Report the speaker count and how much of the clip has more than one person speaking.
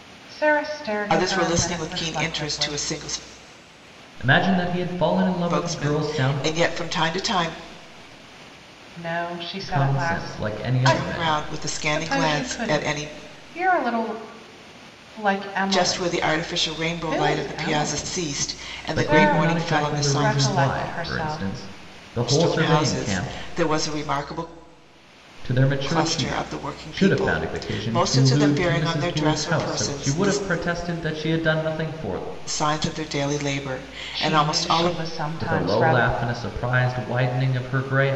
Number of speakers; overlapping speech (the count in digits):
3, about 51%